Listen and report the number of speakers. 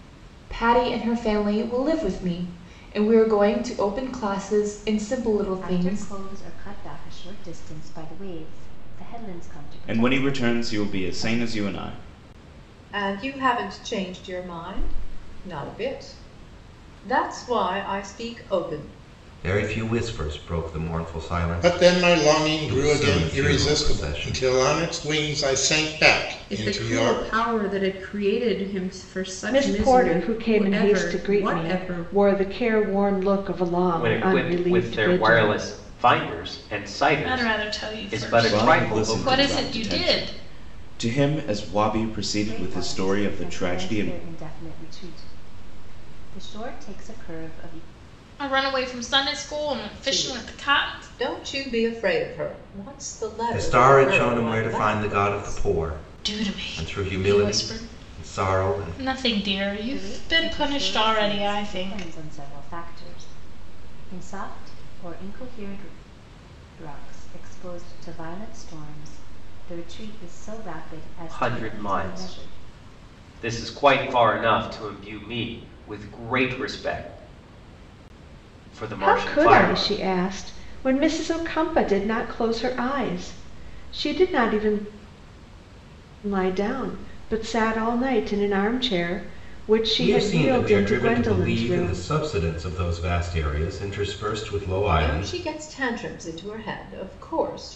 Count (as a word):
ten